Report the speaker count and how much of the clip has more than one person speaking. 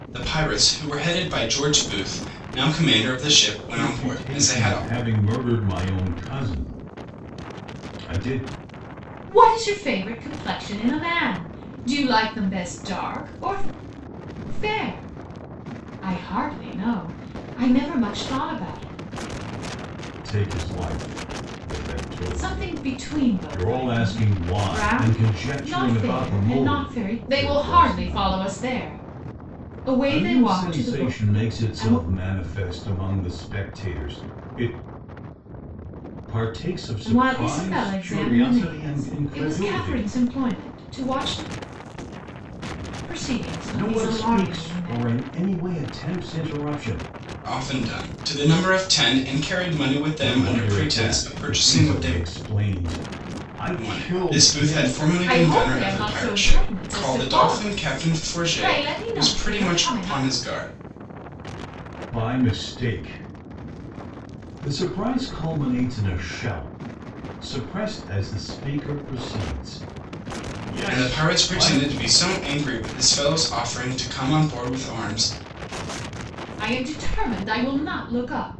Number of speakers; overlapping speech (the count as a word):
three, about 29%